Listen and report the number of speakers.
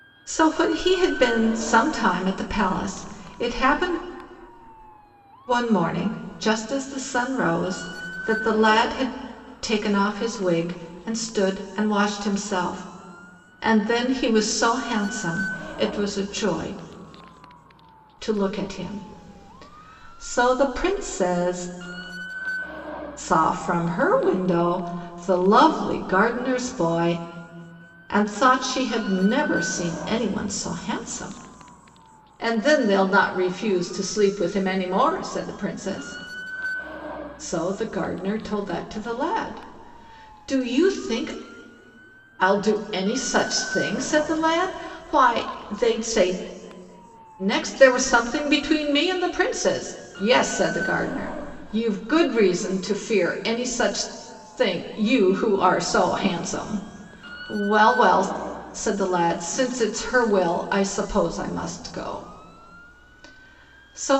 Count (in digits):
1